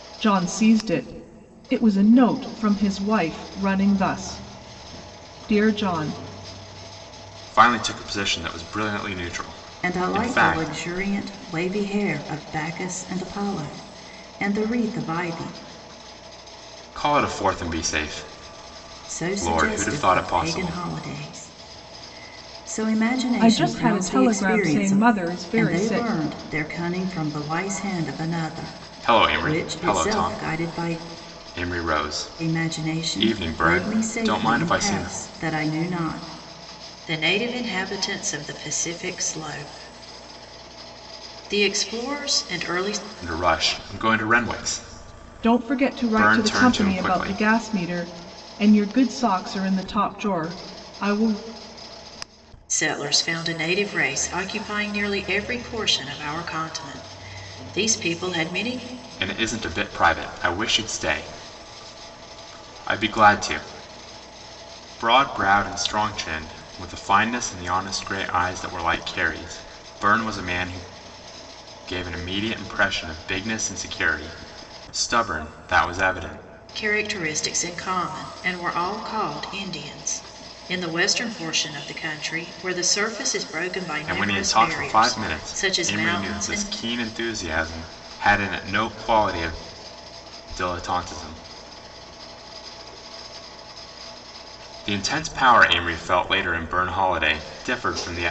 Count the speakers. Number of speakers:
3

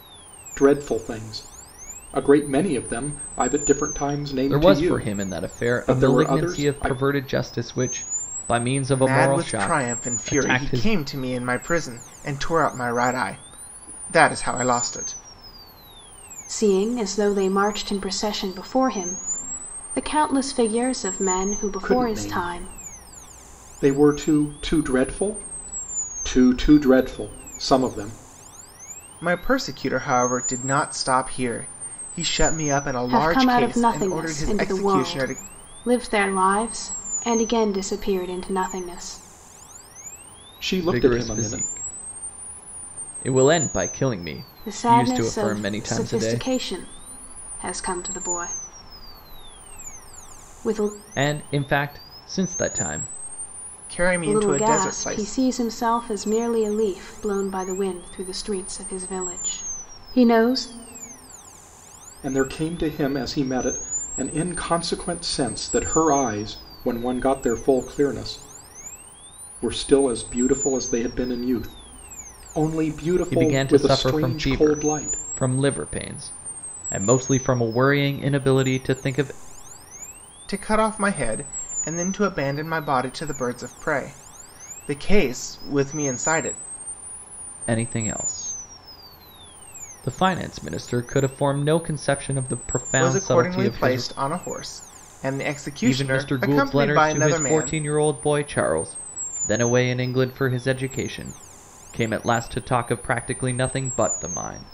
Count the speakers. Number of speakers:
4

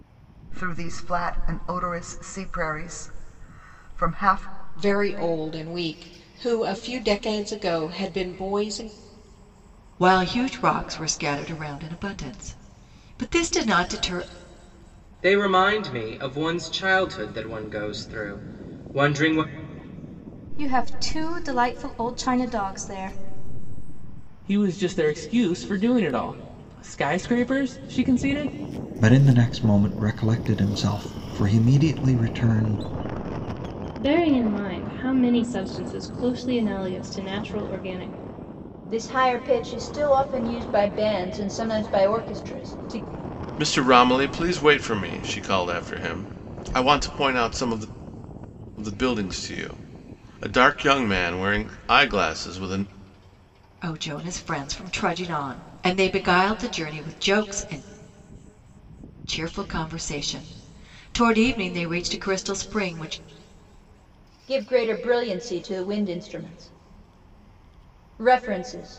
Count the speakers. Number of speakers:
10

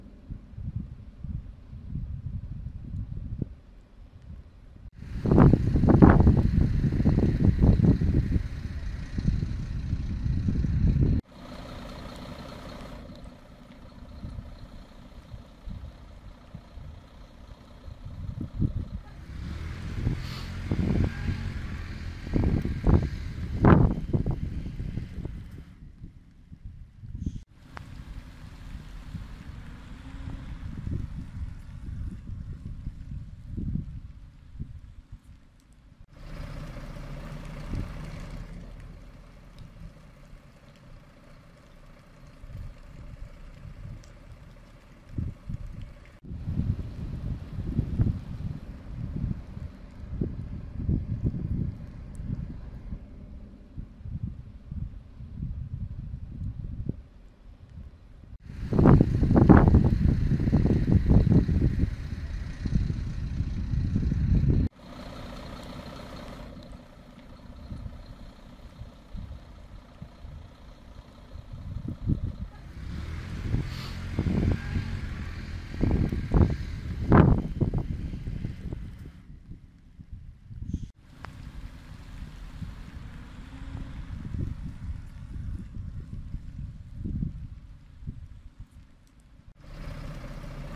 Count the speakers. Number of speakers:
0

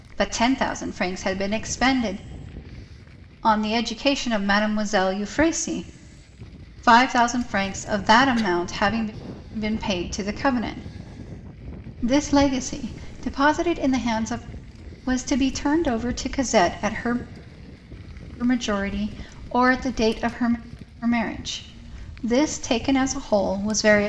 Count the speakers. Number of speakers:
1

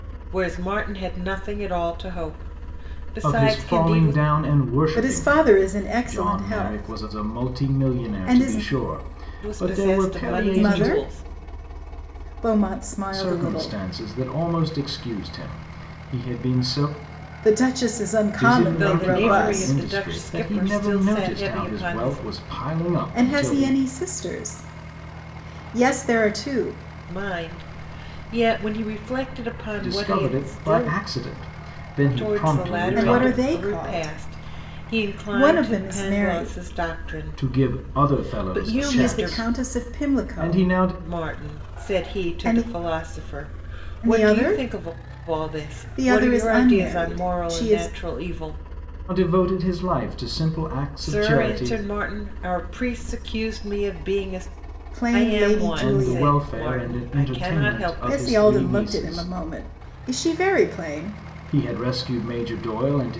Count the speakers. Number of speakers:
3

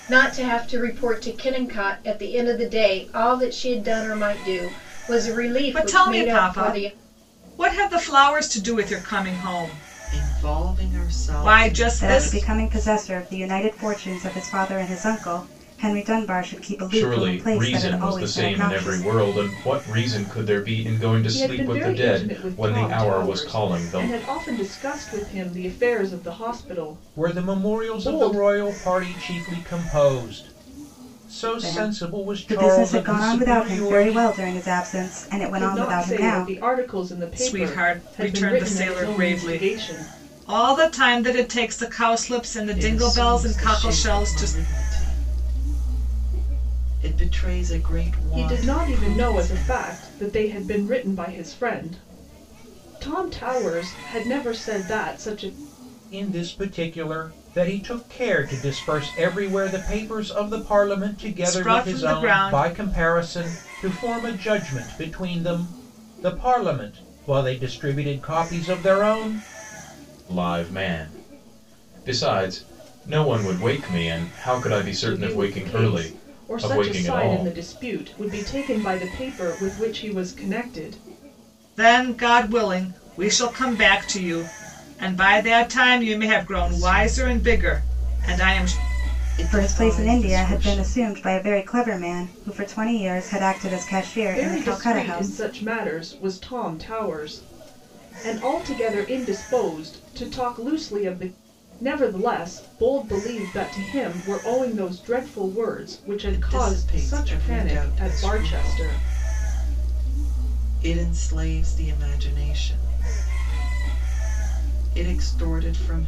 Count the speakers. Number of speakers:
7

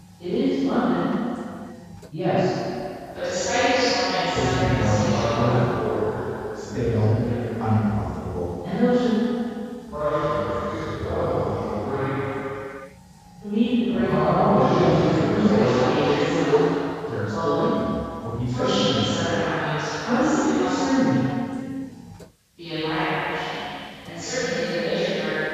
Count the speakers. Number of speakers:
4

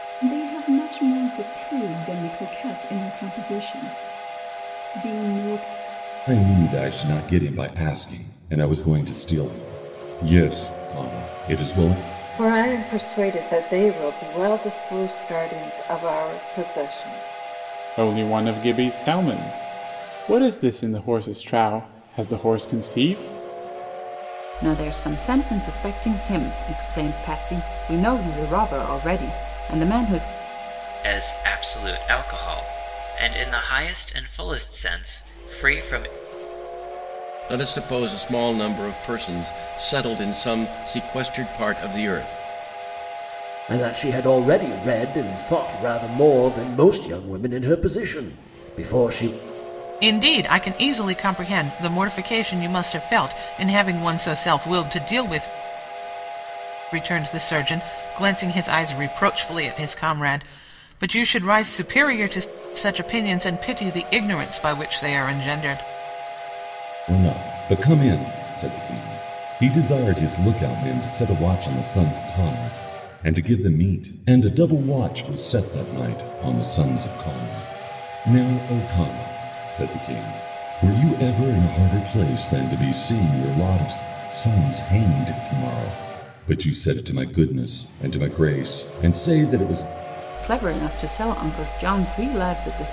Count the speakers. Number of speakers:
9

